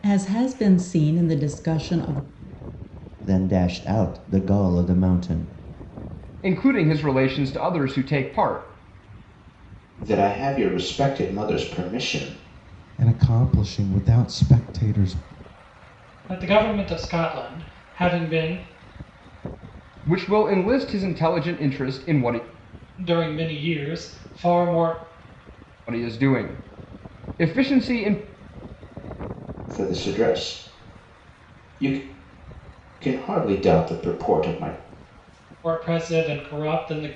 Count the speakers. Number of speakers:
six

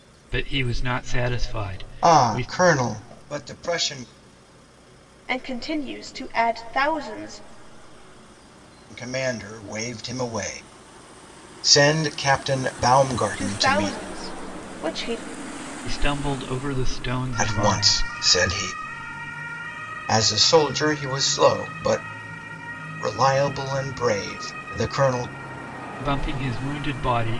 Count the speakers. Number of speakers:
three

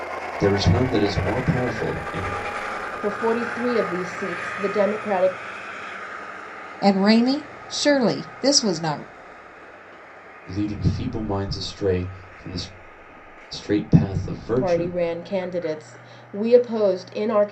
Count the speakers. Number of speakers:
three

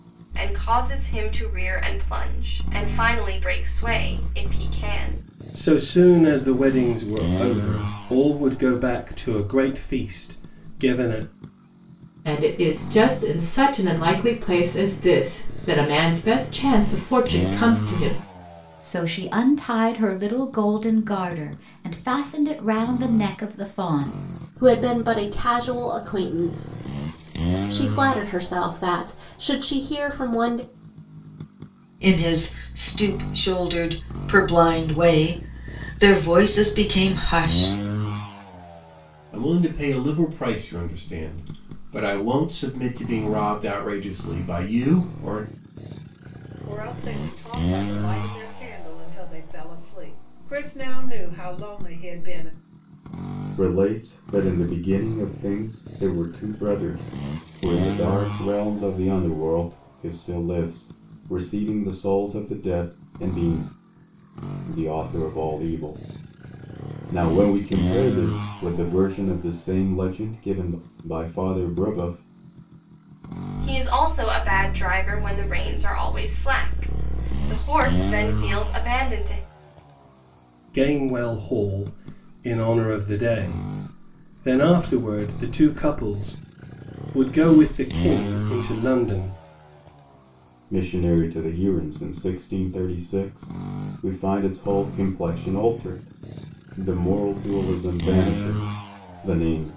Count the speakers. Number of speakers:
nine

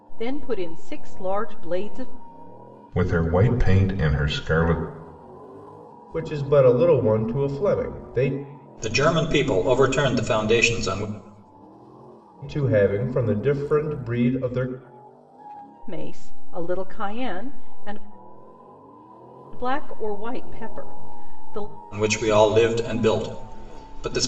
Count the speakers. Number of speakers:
four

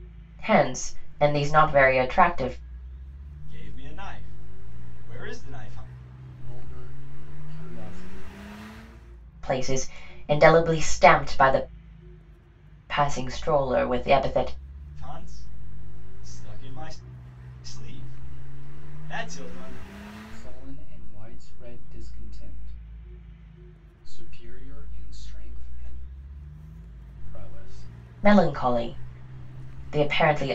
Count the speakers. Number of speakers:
three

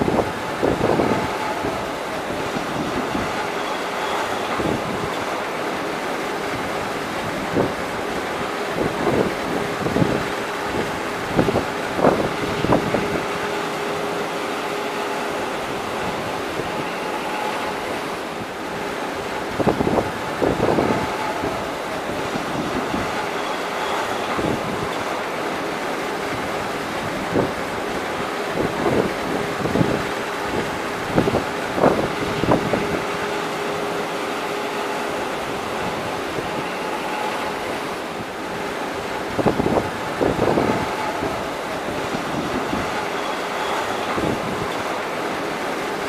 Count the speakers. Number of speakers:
zero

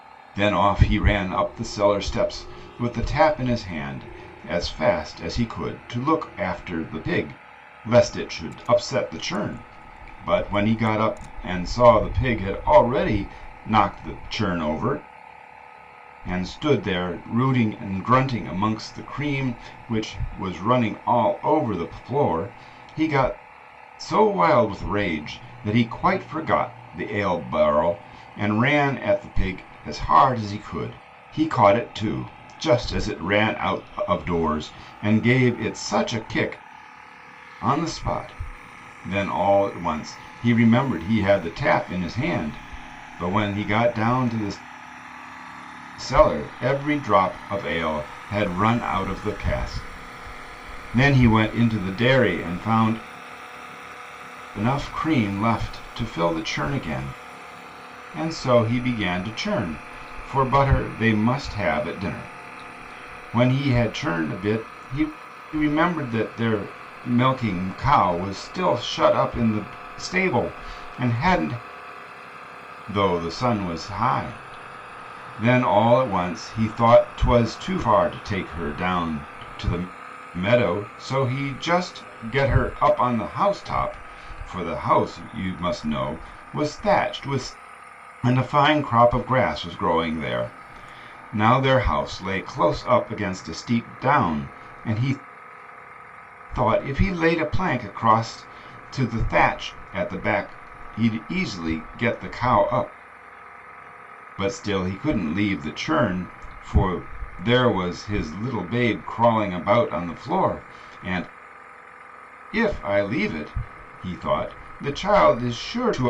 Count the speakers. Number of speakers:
one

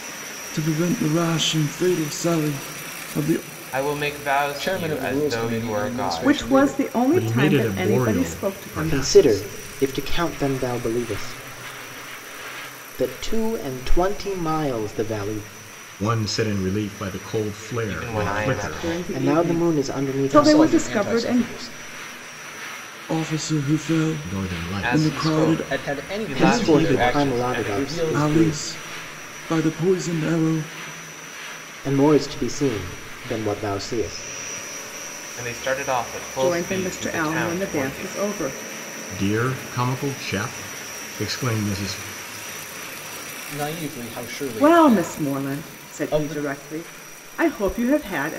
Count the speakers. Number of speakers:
six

